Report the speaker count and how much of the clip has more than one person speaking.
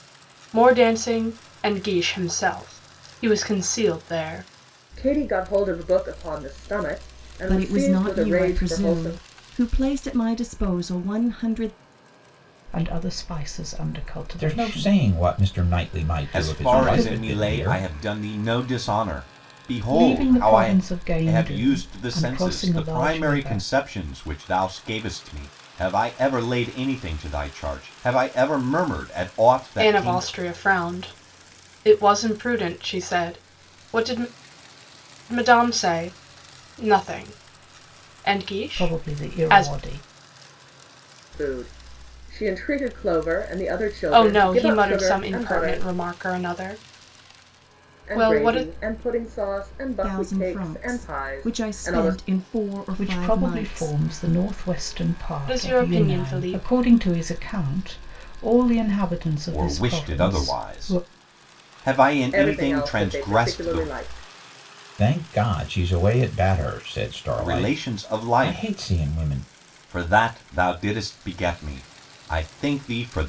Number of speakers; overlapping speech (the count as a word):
six, about 31%